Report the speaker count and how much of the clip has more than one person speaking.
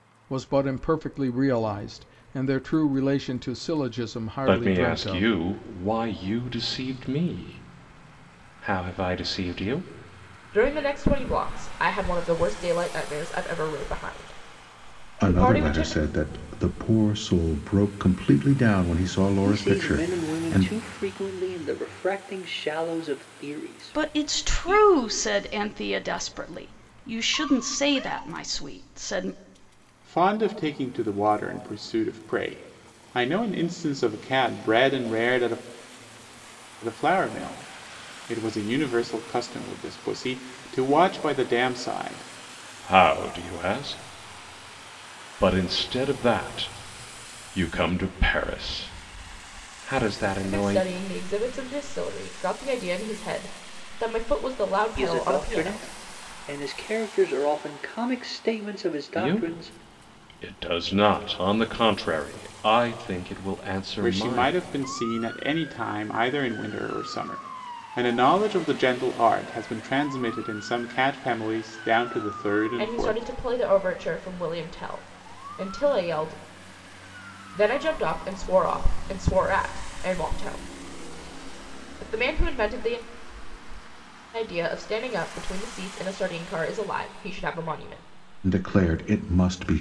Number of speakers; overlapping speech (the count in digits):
7, about 8%